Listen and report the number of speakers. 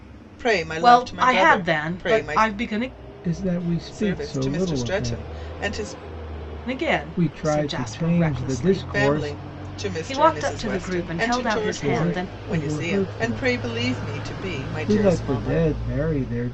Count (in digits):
3